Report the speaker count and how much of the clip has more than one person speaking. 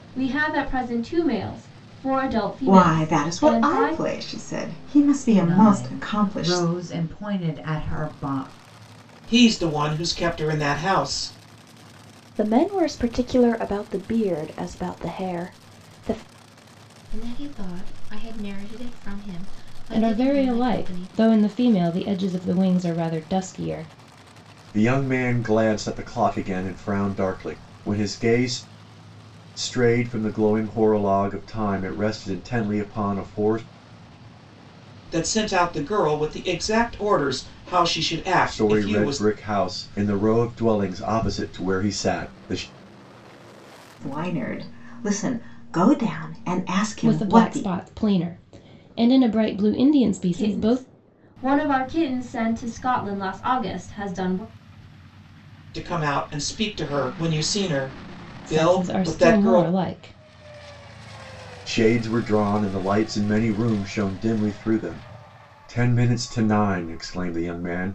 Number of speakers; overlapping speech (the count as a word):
eight, about 11%